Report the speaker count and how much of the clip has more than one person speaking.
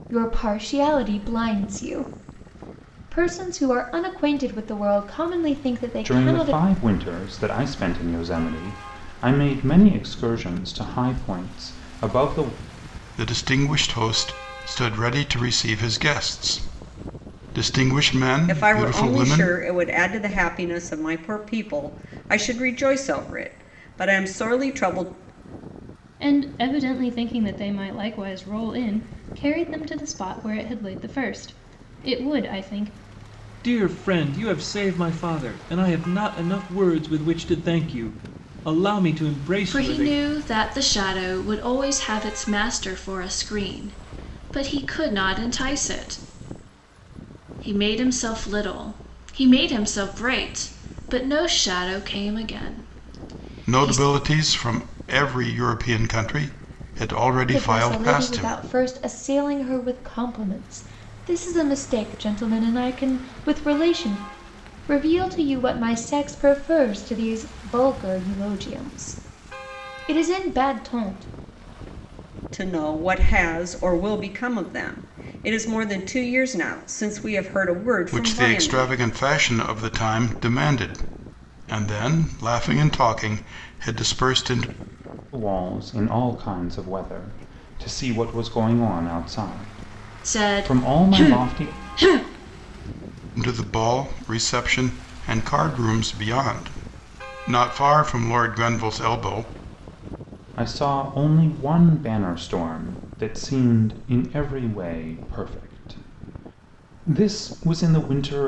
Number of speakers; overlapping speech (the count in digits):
7, about 6%